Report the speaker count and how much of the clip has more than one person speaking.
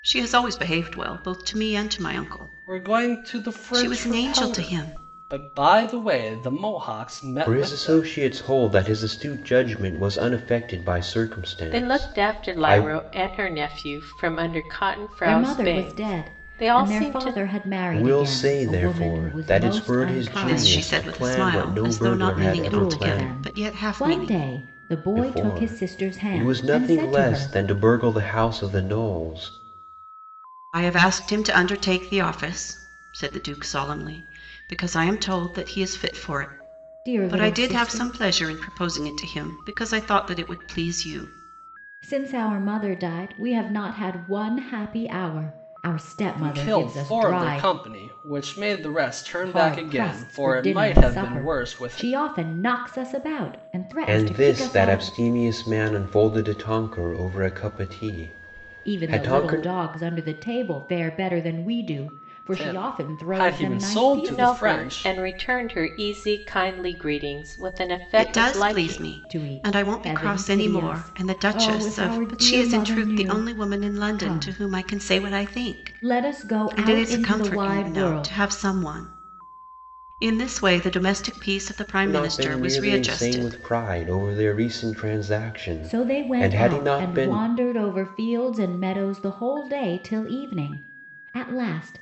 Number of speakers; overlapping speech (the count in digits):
5, about 40%